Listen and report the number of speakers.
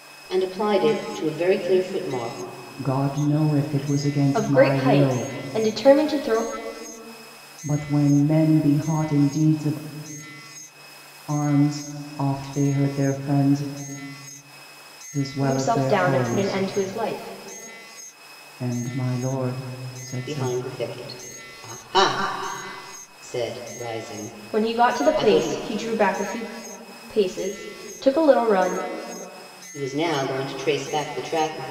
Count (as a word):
three